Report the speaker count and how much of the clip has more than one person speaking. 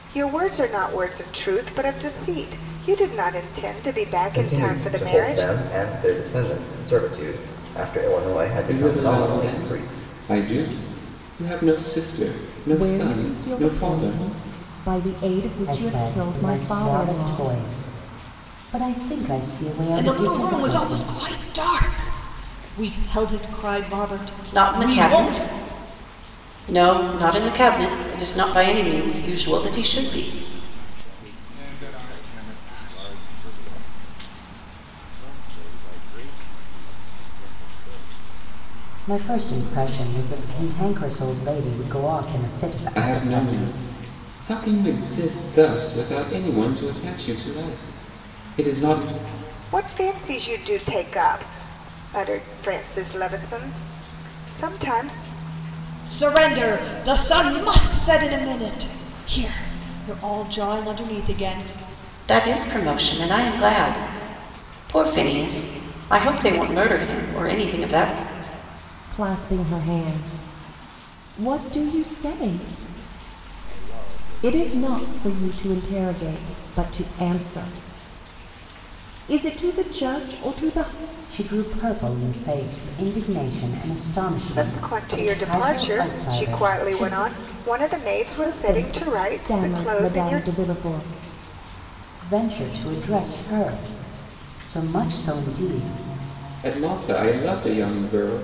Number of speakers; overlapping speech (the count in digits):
9, about 22%